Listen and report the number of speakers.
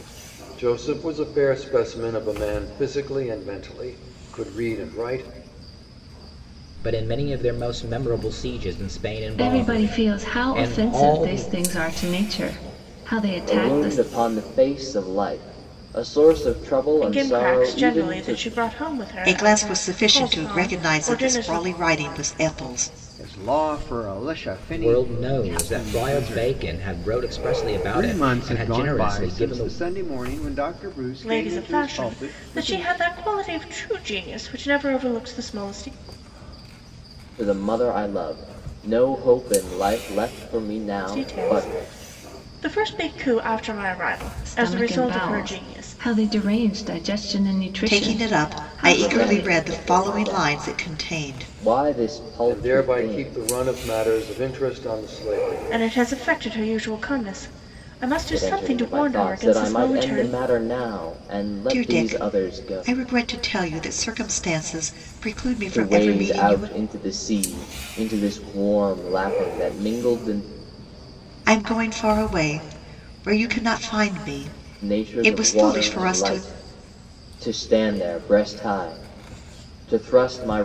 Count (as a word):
seven